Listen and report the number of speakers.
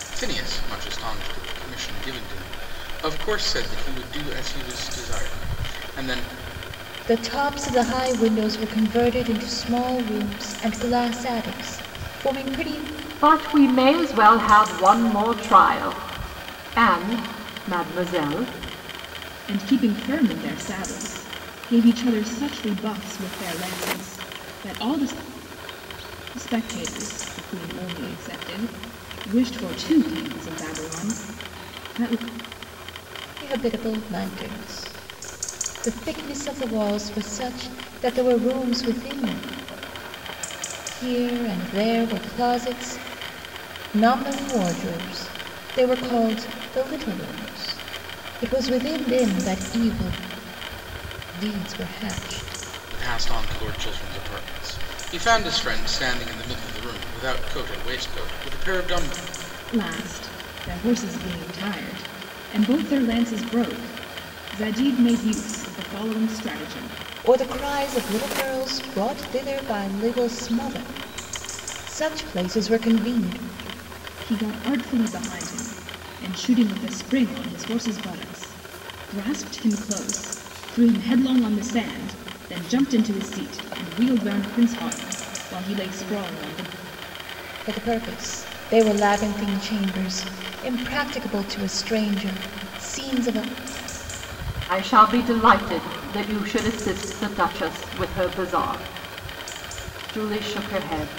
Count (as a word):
four